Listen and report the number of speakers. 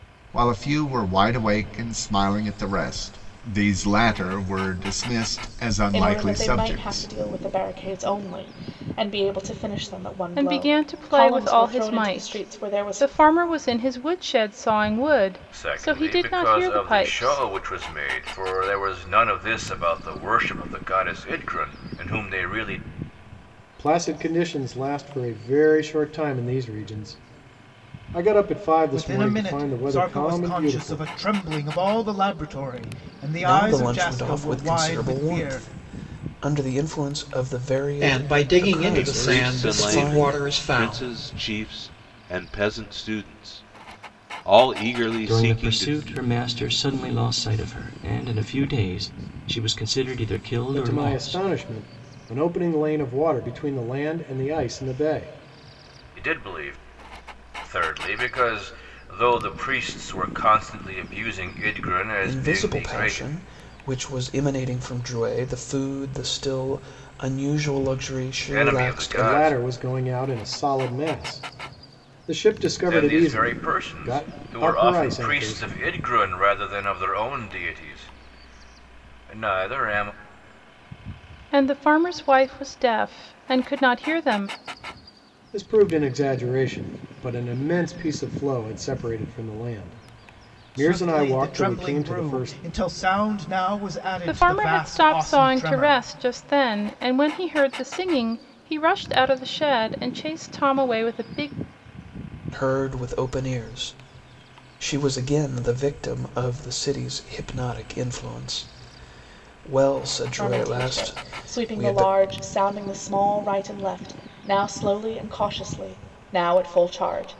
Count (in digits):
10